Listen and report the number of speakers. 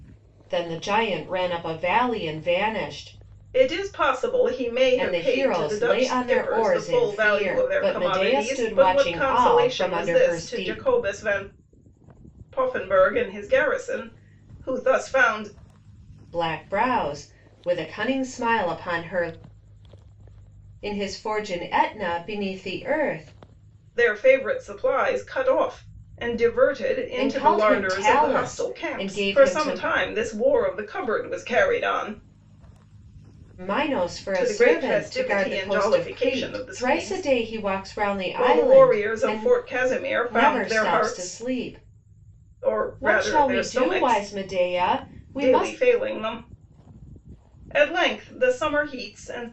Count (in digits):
2